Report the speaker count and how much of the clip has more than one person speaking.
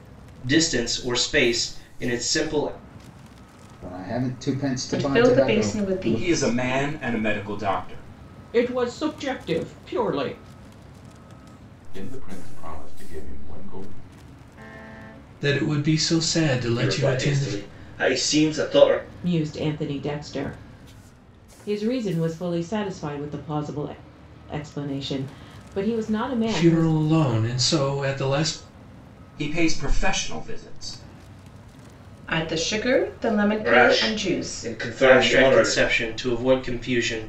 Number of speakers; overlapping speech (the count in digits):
8, about 13%